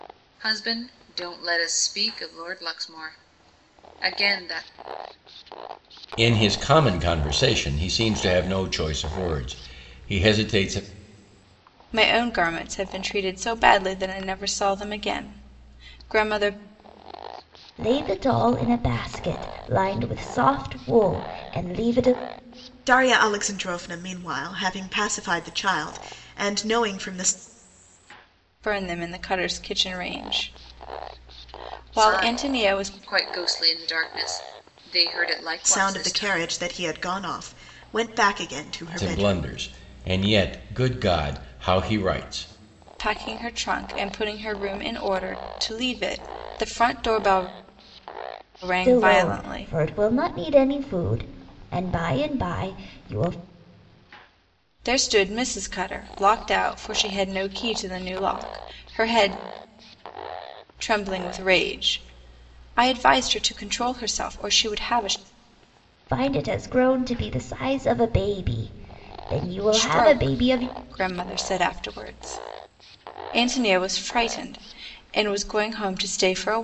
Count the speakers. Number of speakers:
5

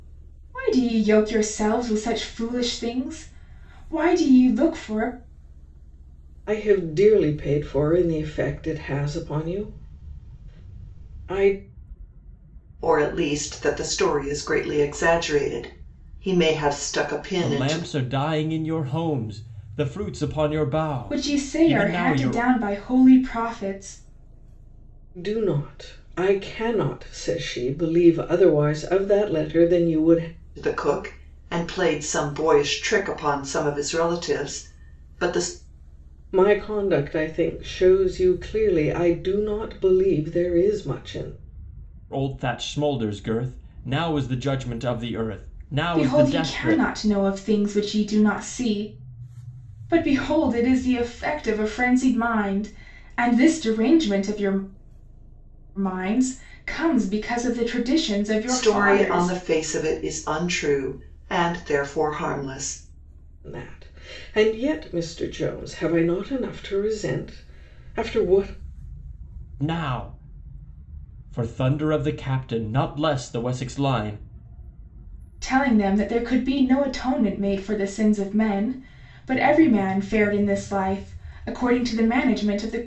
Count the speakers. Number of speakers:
4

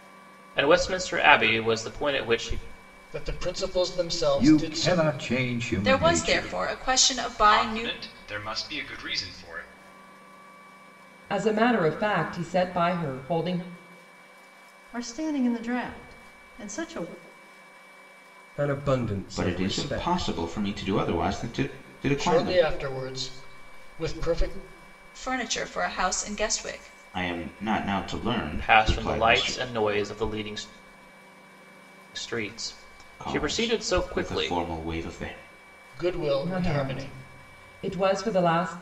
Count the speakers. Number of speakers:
9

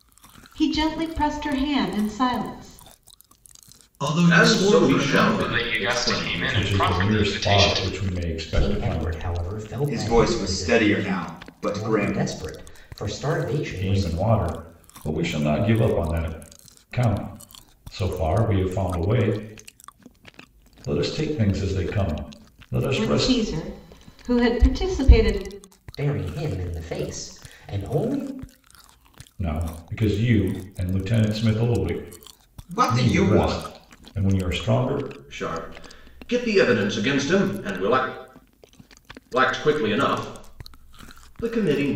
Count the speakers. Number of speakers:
7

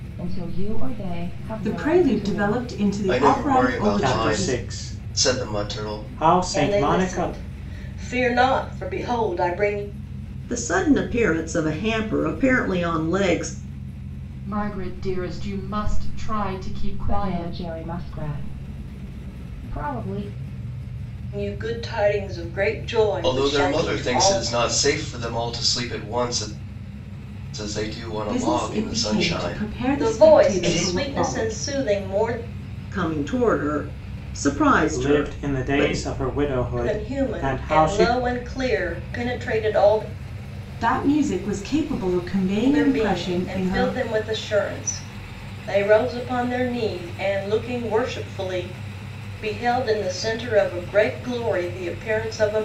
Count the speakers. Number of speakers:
7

